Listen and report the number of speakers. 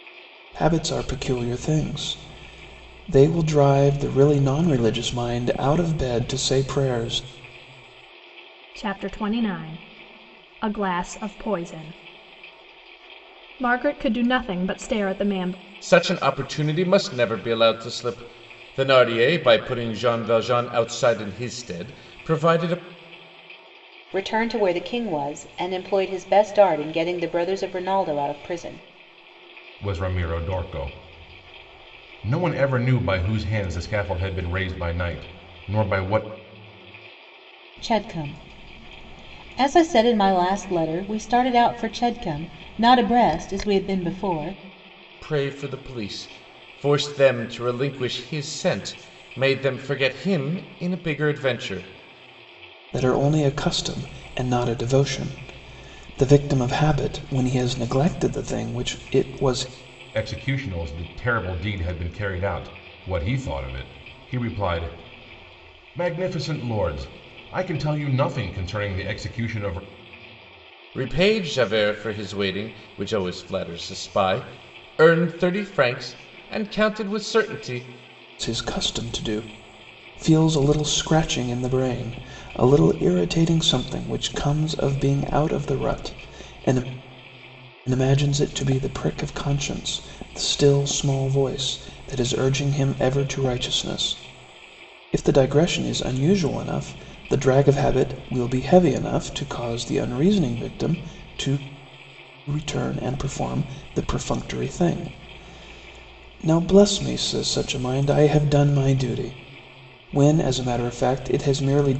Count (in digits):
5